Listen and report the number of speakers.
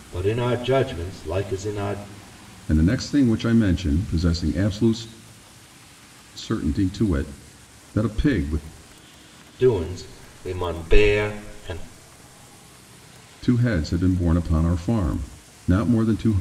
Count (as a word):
two